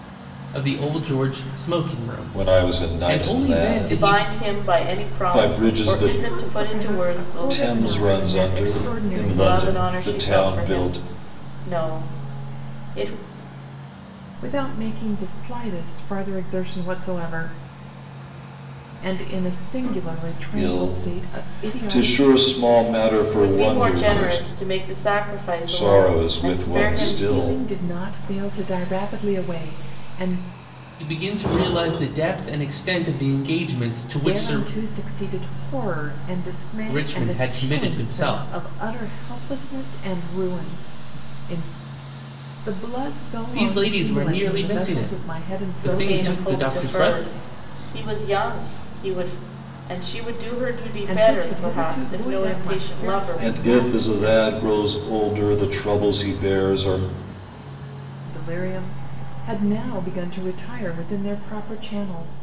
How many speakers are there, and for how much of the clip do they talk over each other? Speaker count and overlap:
4, about 37%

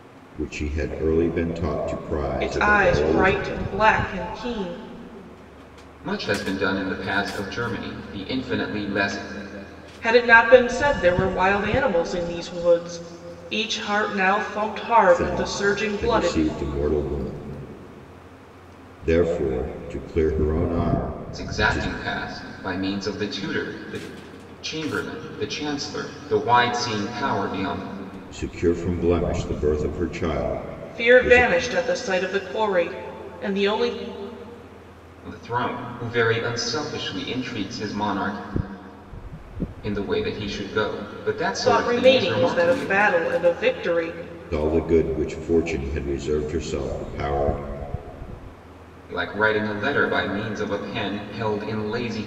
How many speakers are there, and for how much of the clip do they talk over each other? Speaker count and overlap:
3, about 9%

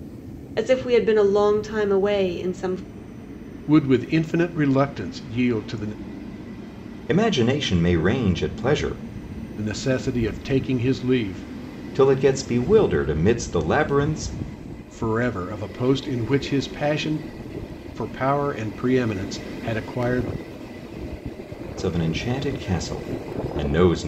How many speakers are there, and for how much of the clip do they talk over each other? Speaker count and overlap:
3, no overlap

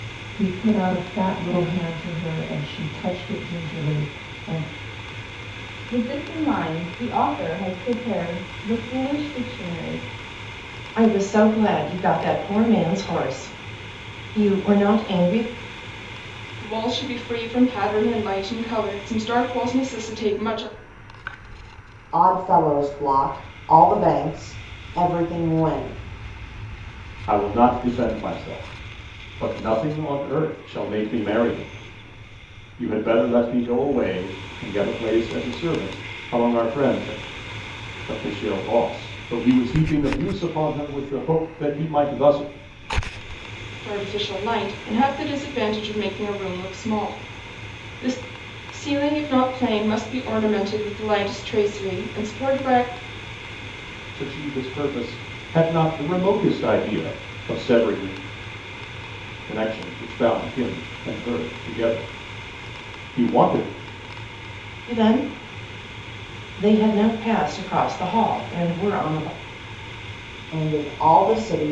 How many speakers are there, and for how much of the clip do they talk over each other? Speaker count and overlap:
6, no overlap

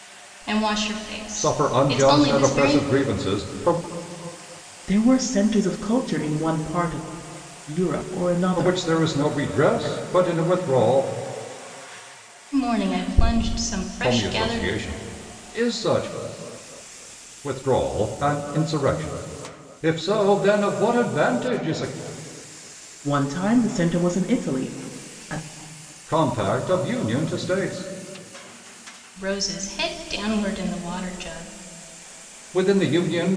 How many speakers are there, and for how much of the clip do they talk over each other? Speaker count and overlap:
3, about 11%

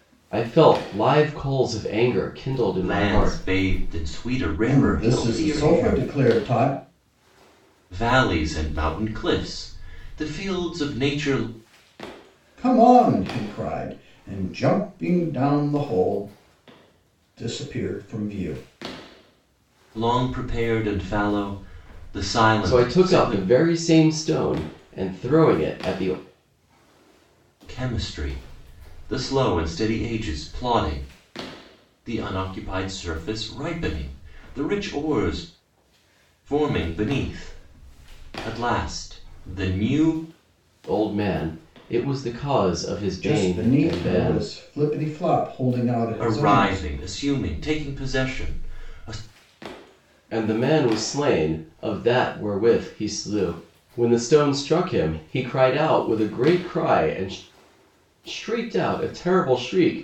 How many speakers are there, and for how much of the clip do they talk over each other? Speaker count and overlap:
3, about 8%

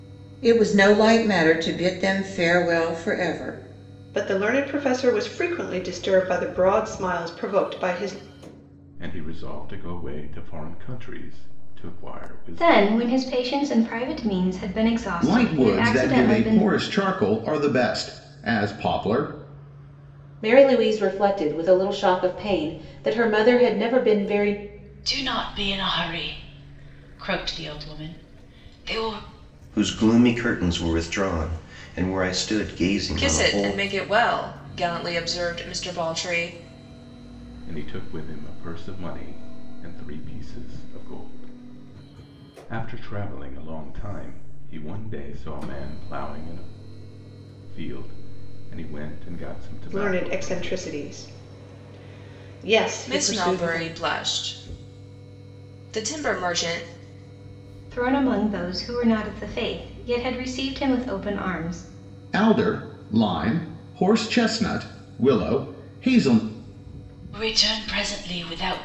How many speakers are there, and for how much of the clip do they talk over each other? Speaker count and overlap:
9, about 6%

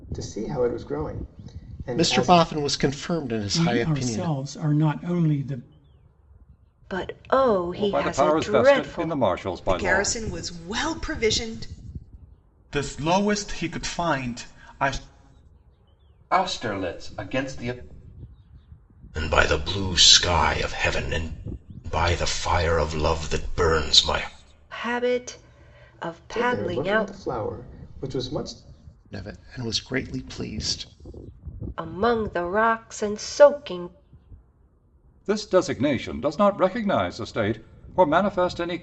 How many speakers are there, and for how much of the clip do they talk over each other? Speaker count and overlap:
9, about 11%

